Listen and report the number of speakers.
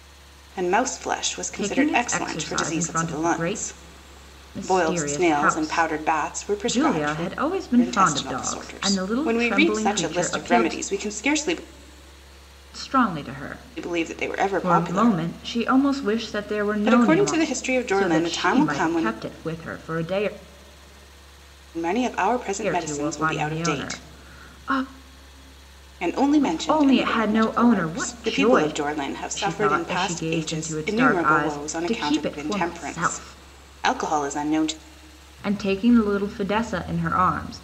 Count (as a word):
two